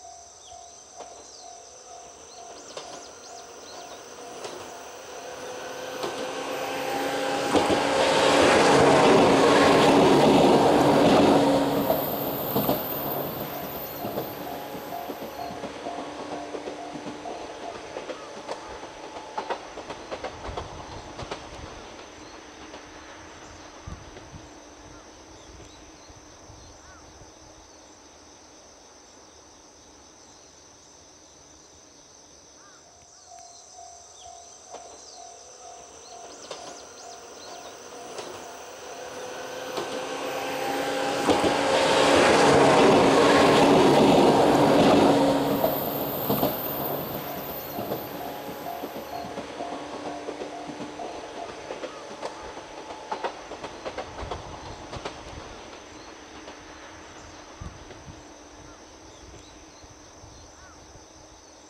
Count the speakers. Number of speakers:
zero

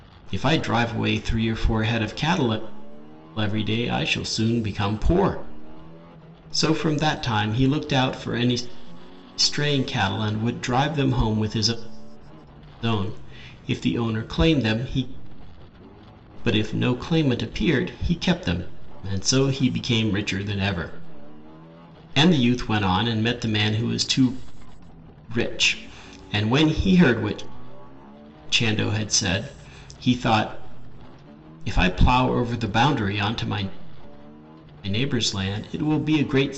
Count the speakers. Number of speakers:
one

